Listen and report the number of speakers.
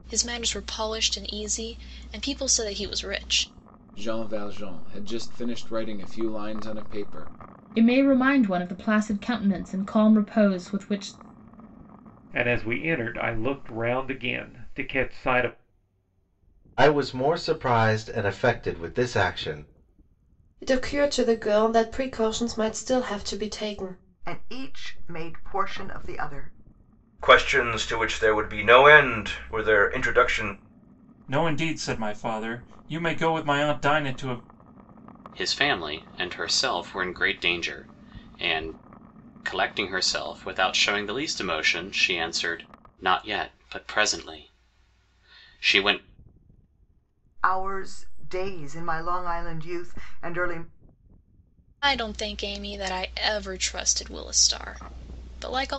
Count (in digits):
10